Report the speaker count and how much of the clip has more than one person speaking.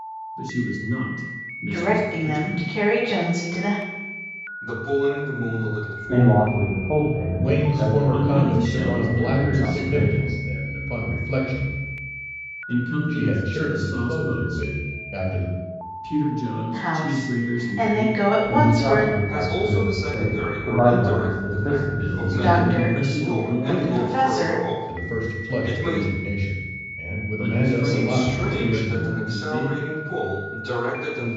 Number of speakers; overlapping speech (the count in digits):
5, about 55%